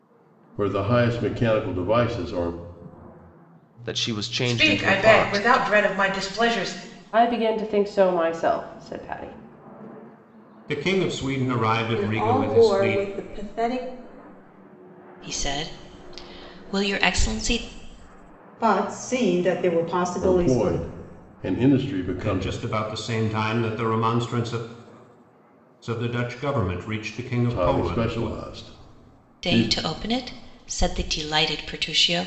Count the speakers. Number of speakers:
8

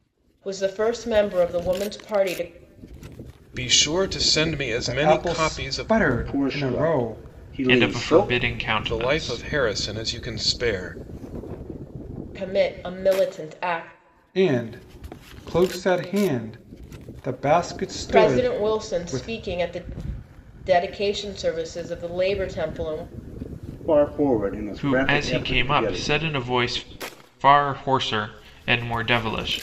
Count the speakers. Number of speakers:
5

